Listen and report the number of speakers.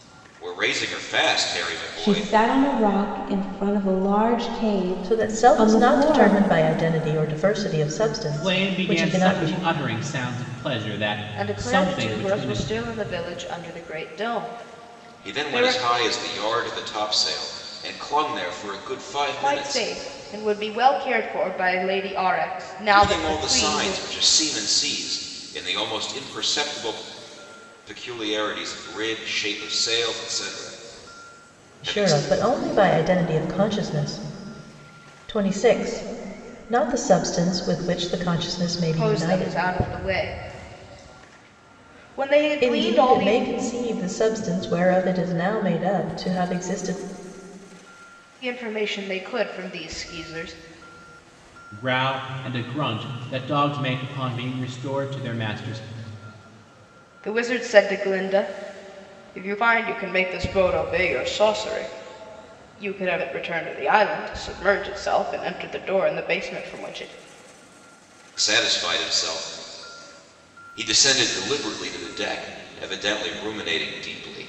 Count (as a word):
five